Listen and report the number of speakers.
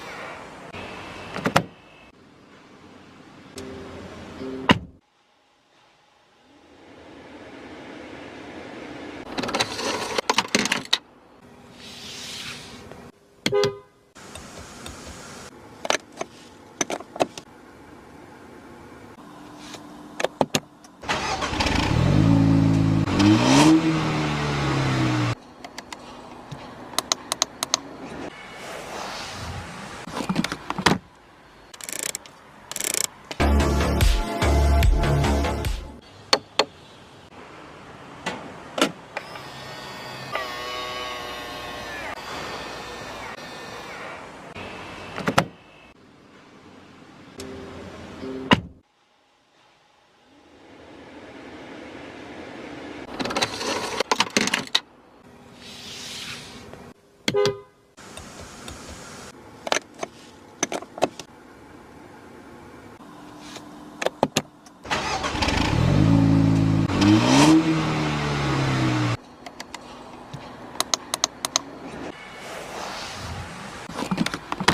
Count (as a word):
zero